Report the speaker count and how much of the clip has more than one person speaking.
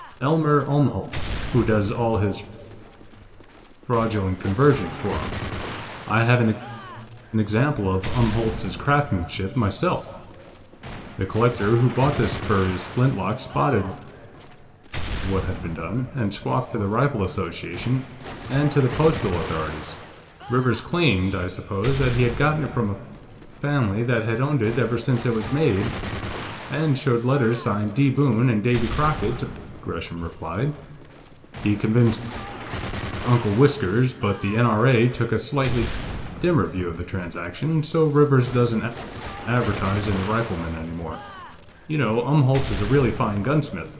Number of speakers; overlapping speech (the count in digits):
1, no overlap